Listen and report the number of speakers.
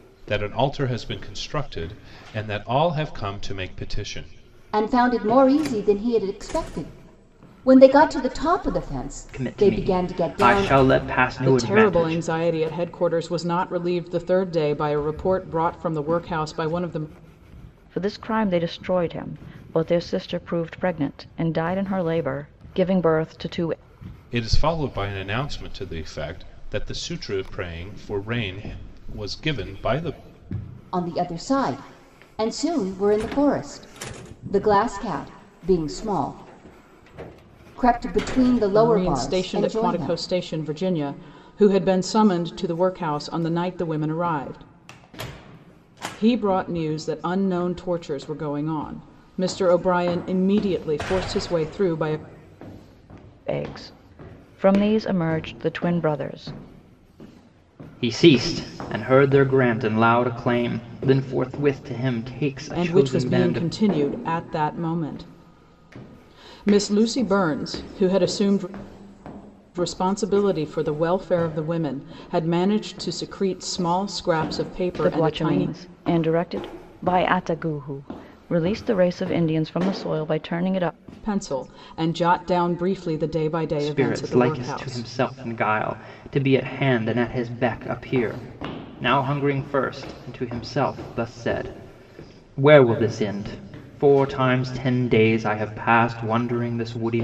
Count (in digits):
5